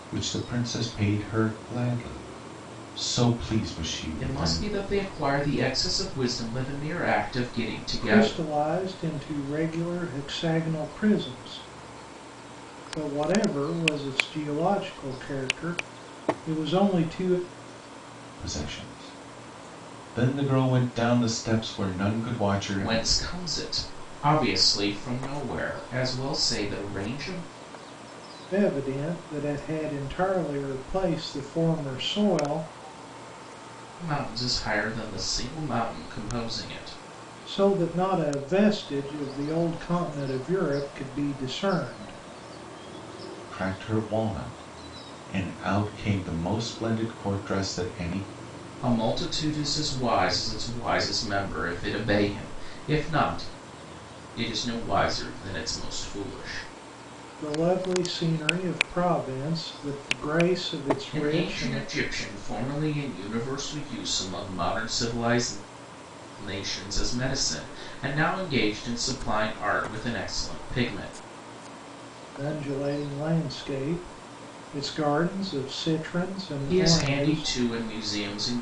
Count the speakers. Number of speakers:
three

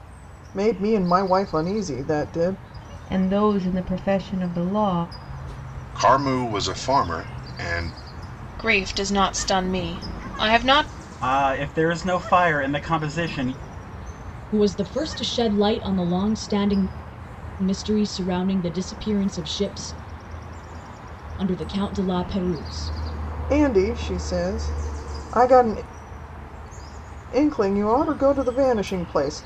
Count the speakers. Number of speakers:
six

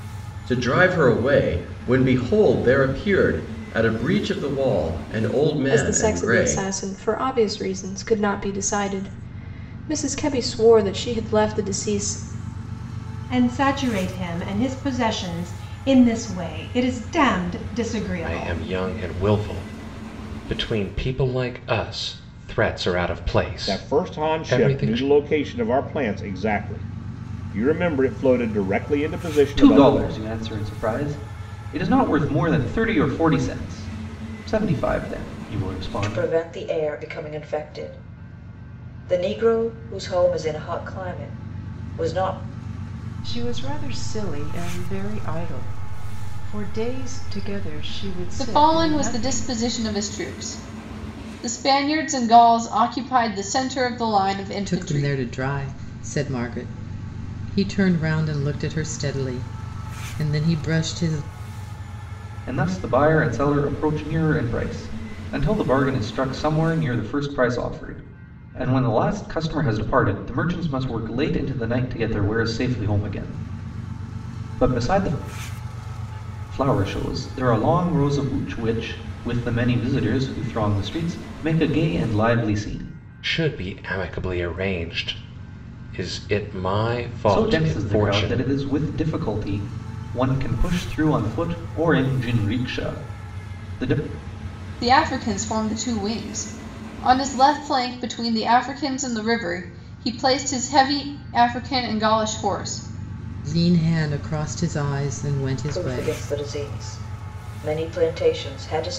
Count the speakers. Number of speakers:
ten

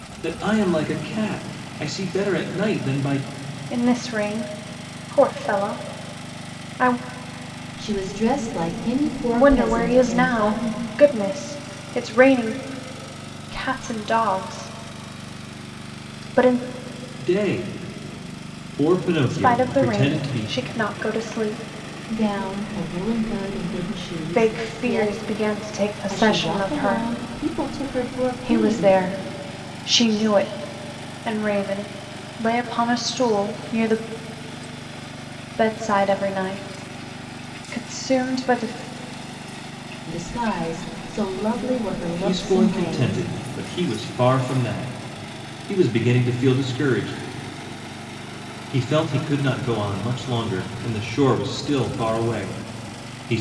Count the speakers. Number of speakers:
three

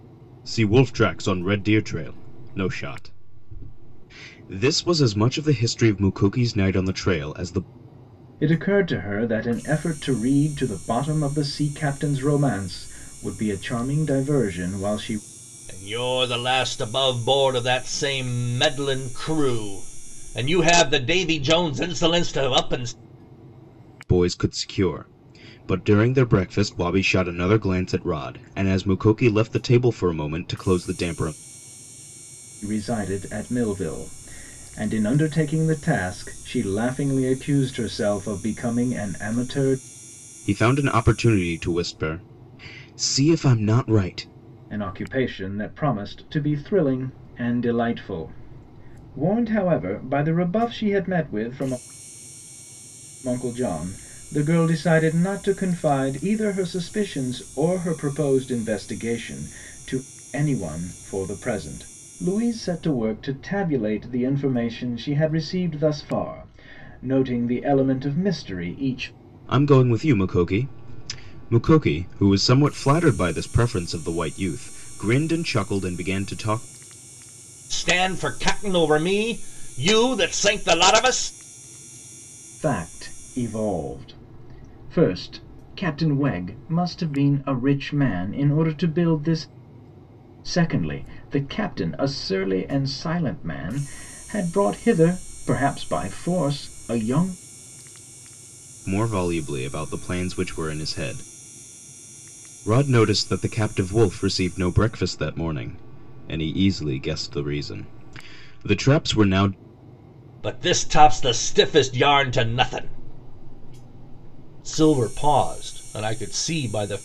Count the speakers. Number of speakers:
three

